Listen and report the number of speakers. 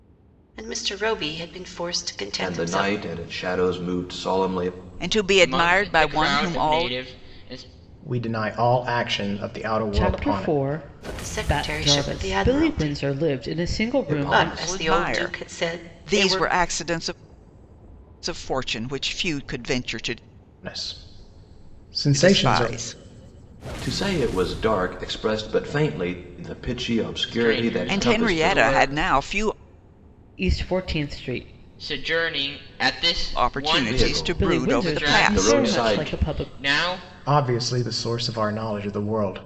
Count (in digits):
6